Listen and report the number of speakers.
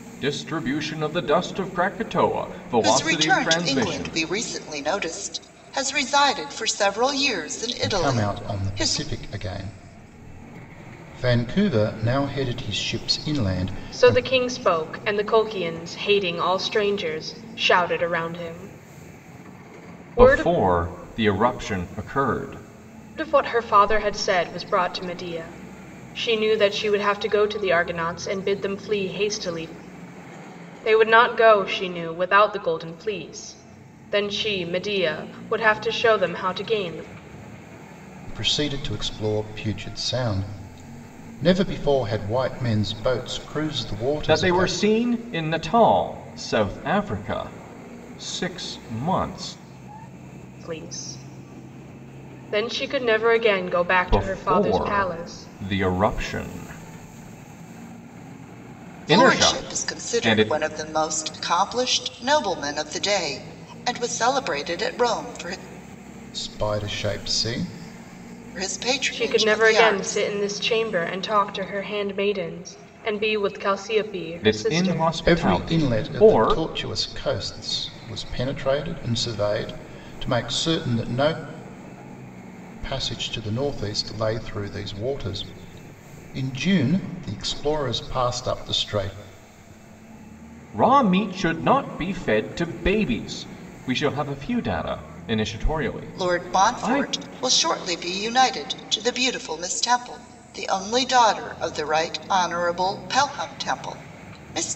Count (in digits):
4